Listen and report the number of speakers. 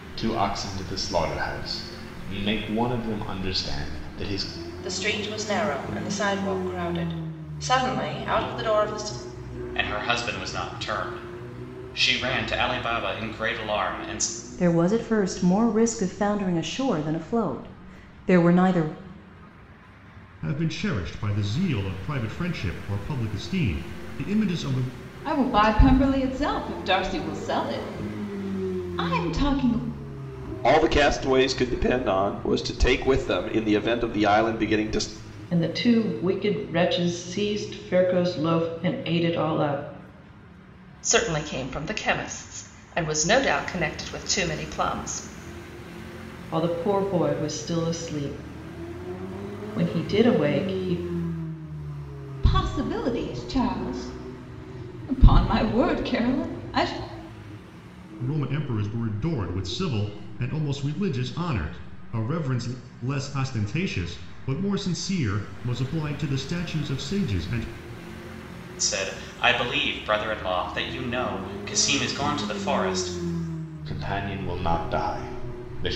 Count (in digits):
9